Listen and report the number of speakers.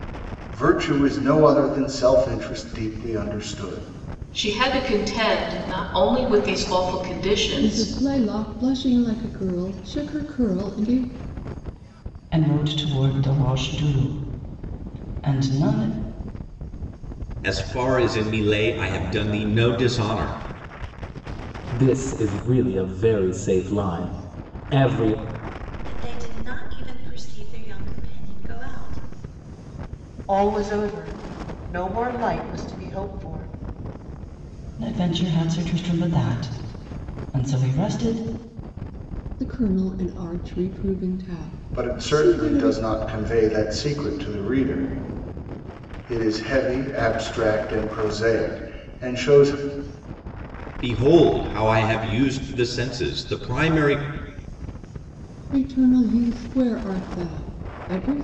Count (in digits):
8